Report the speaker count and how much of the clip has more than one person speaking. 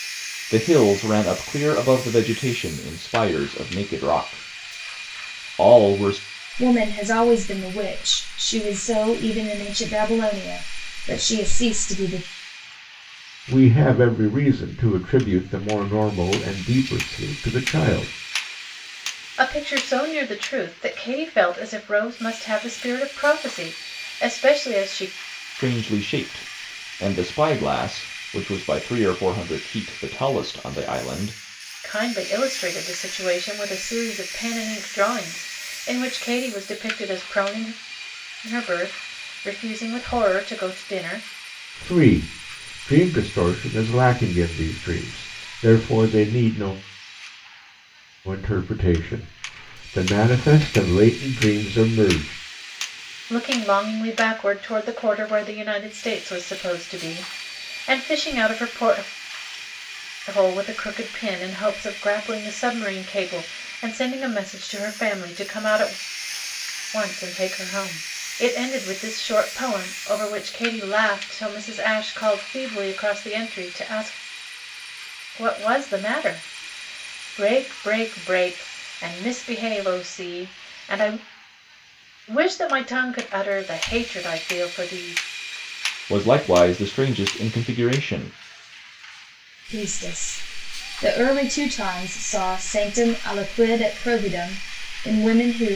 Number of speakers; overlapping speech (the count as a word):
four, no overlap